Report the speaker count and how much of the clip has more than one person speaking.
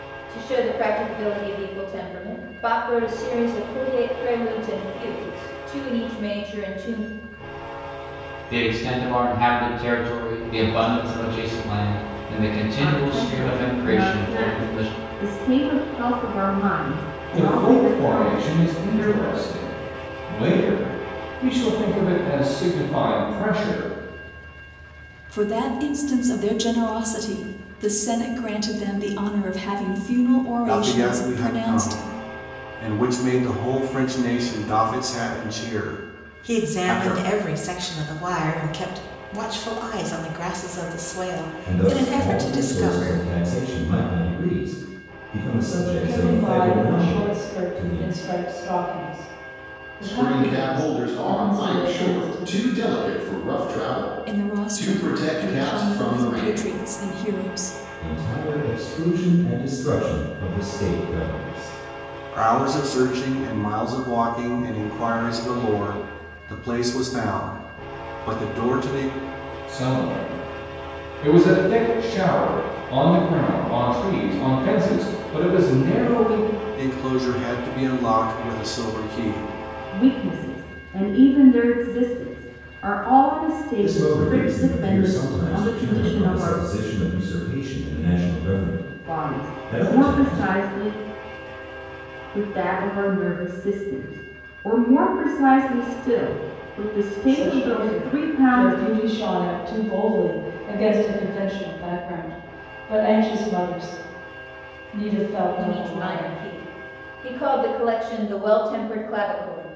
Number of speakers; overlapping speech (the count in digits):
10, about 20%